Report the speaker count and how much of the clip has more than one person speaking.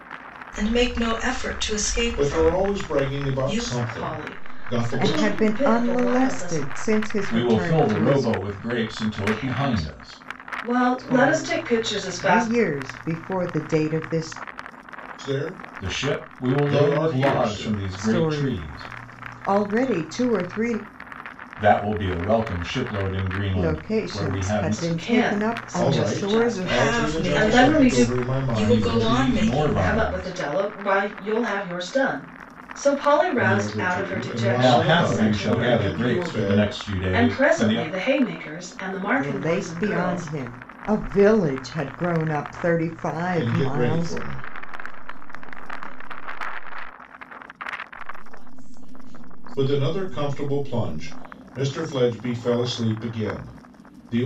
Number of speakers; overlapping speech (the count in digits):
6, about 49%